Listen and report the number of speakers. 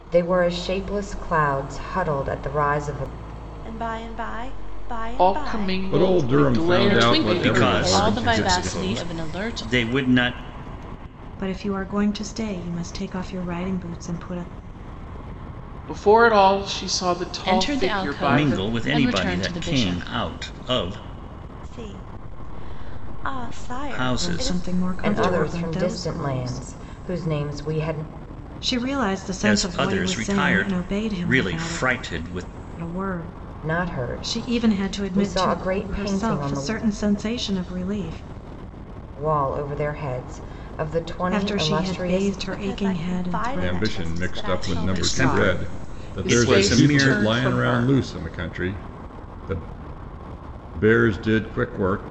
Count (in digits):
7